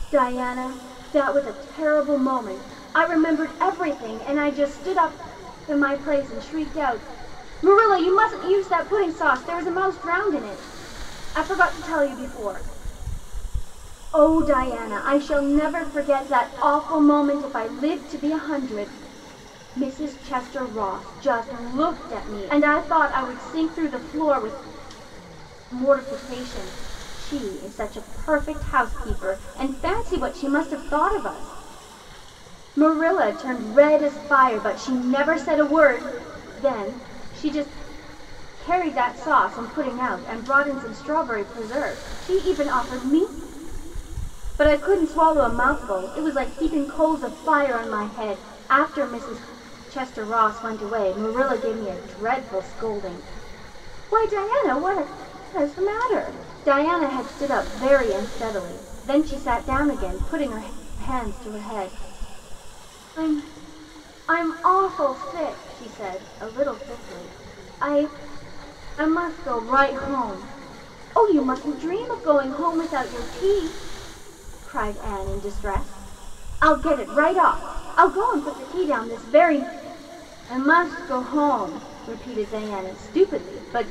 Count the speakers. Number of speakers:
1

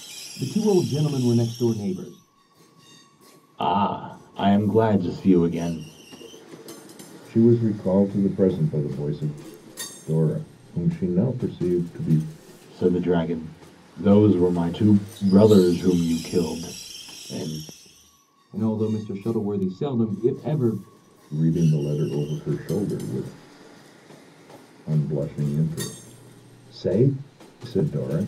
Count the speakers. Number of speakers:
3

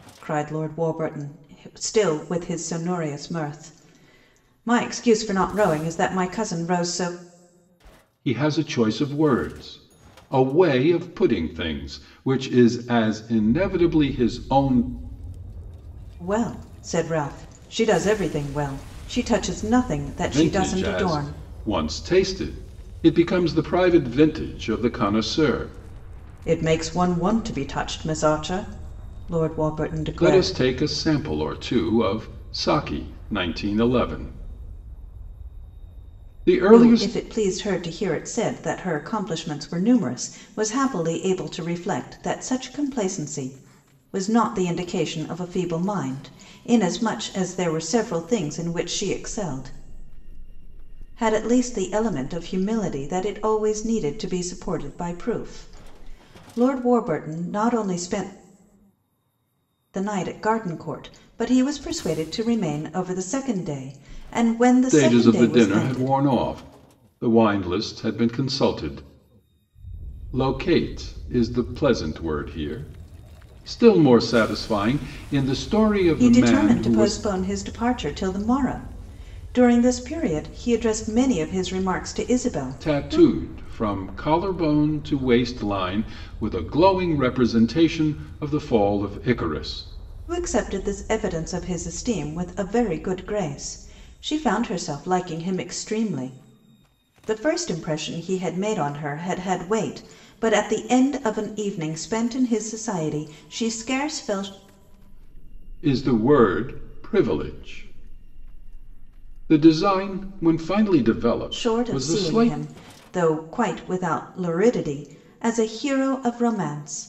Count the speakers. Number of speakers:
2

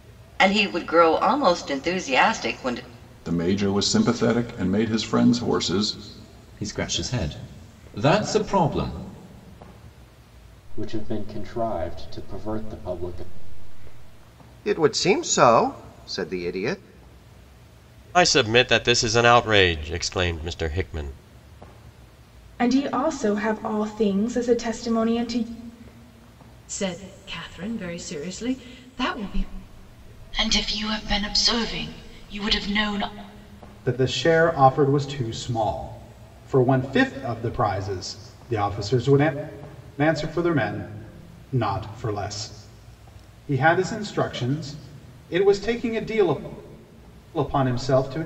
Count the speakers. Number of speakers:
10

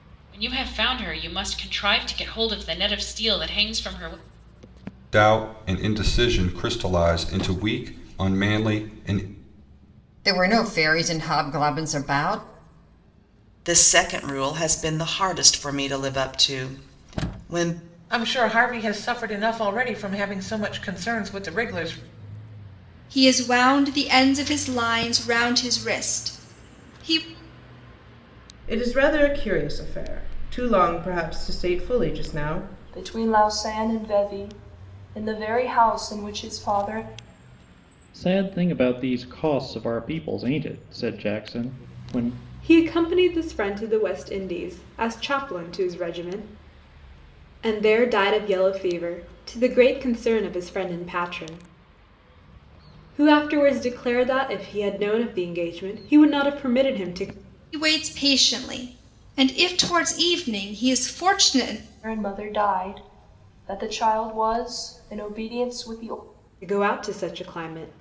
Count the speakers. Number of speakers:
10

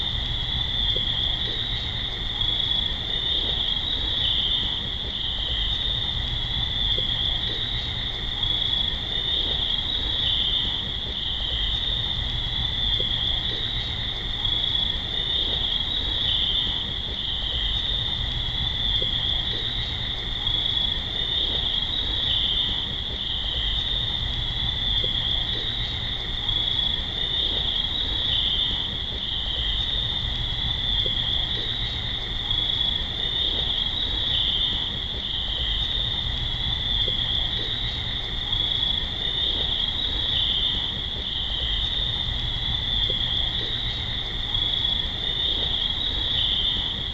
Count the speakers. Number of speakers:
0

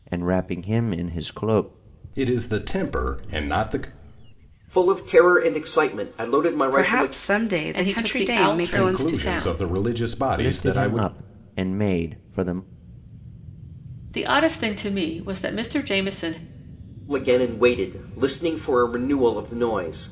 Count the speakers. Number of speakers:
5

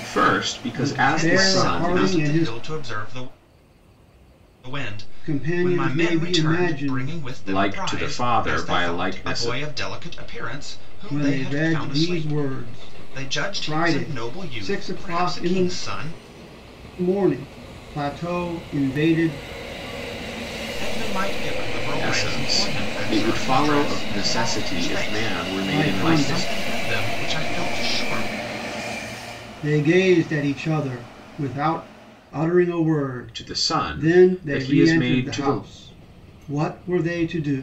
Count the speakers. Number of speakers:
3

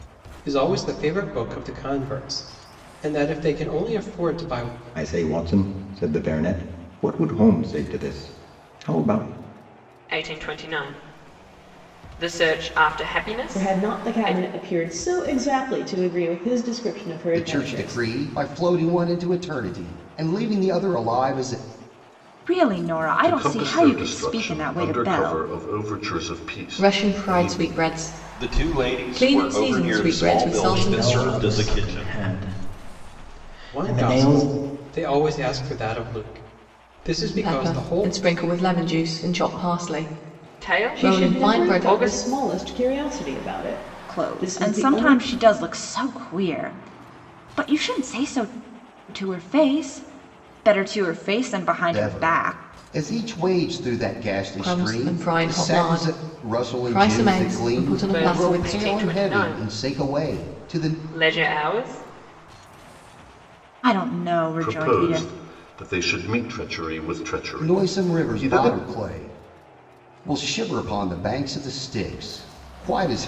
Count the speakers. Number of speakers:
10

